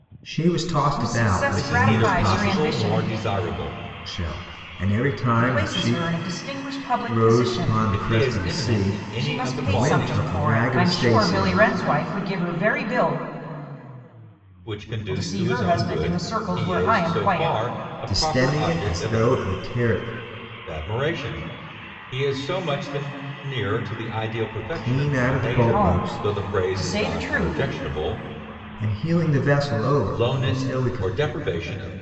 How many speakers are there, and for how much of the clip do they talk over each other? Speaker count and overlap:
three, about 46%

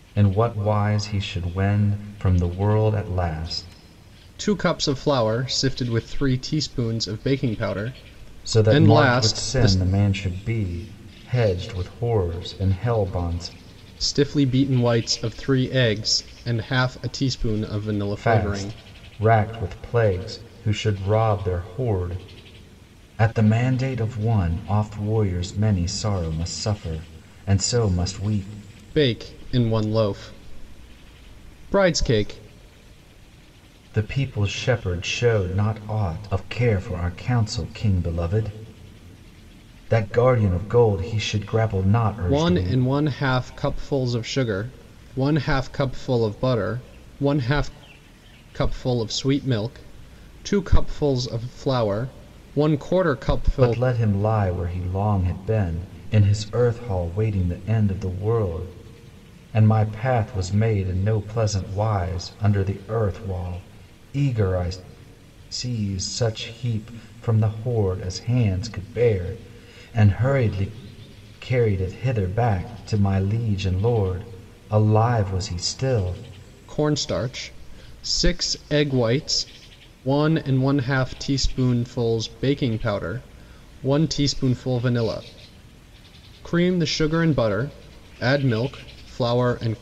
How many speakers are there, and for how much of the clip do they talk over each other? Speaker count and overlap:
two, about 3%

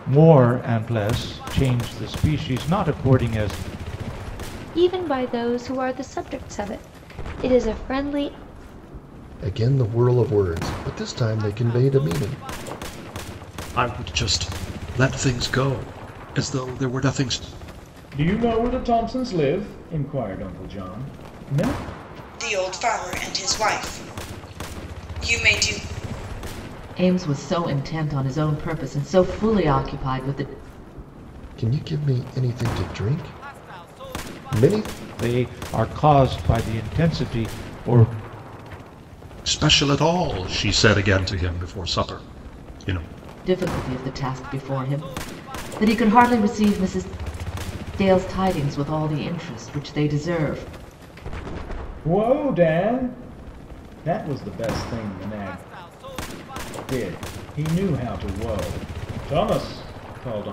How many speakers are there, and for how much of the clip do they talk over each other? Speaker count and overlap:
seven, no overlap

